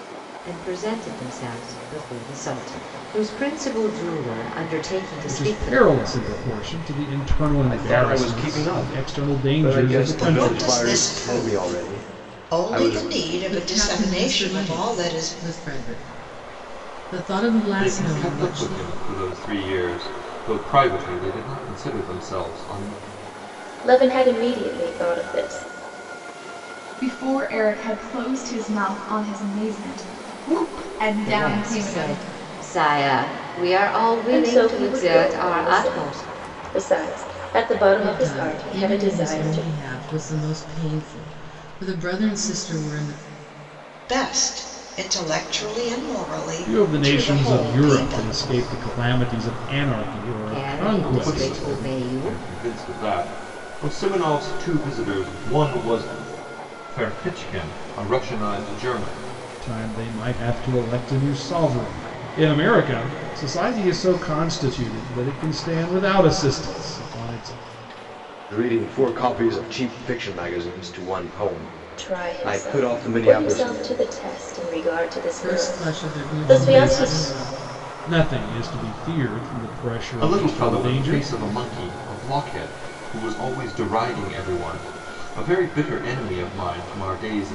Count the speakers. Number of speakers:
eight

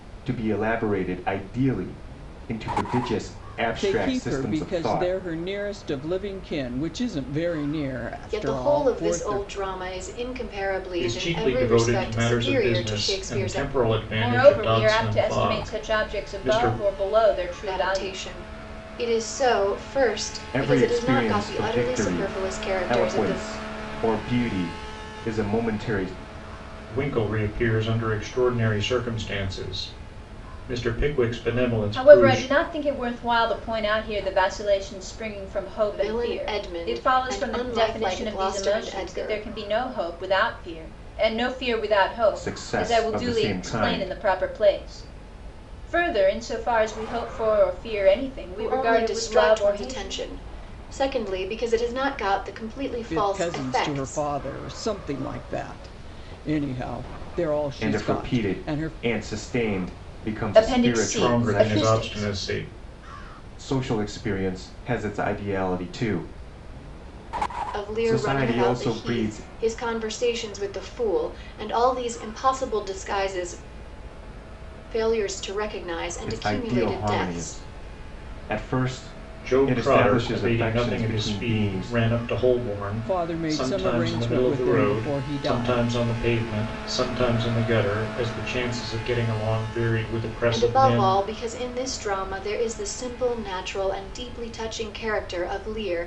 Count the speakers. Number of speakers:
five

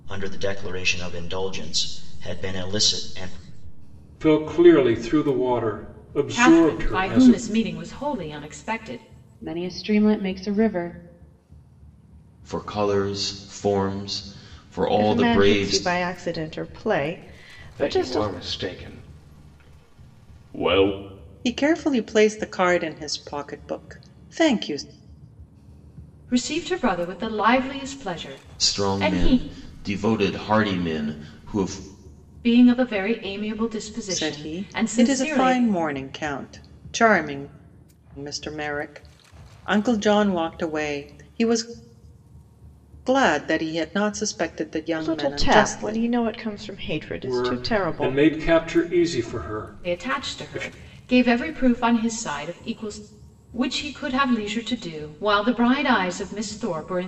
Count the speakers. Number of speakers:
eight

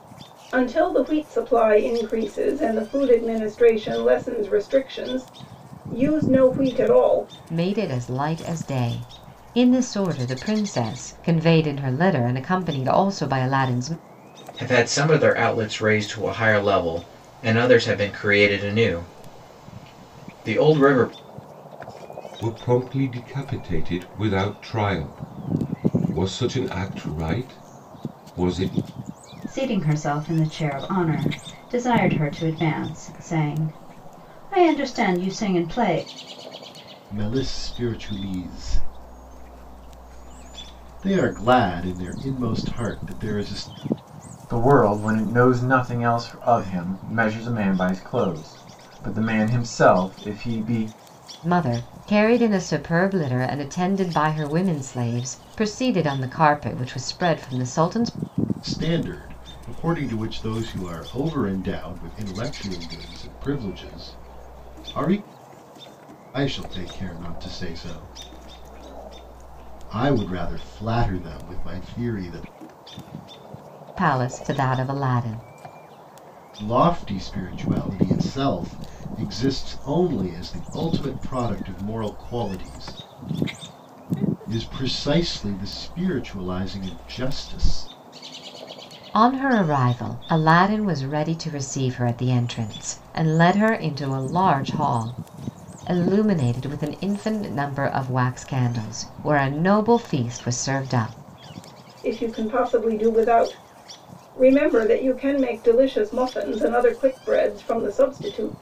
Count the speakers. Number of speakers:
seven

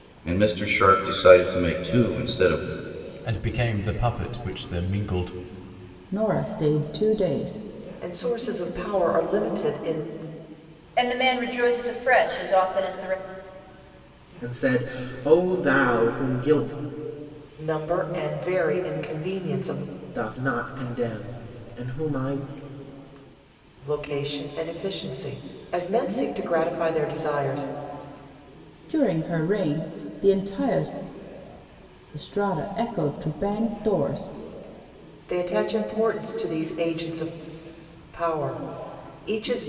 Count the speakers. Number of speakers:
six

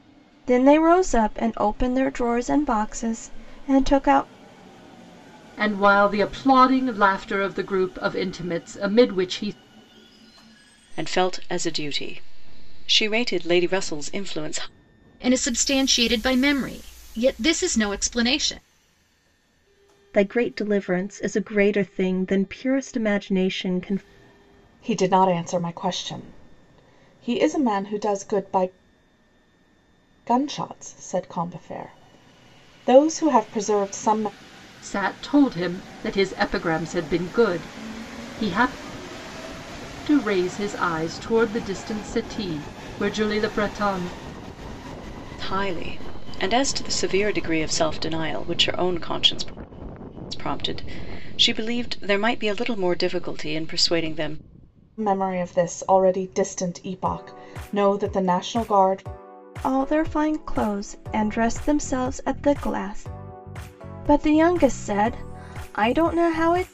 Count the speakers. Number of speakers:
six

